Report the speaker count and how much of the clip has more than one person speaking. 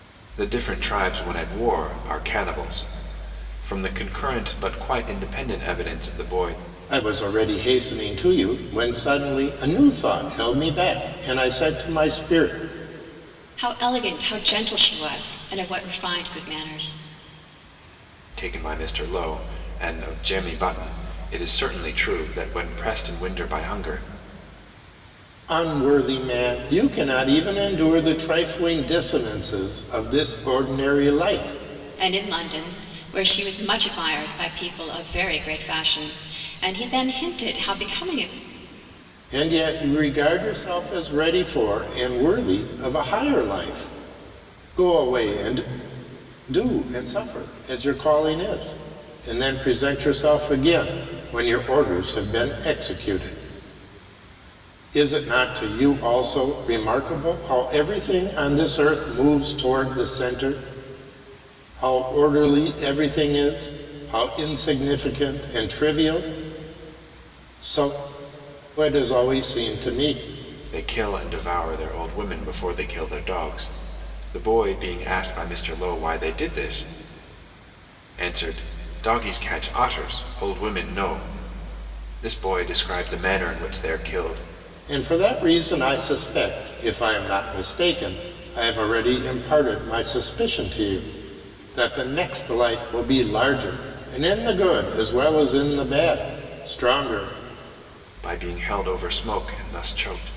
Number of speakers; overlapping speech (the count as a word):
three, no overlap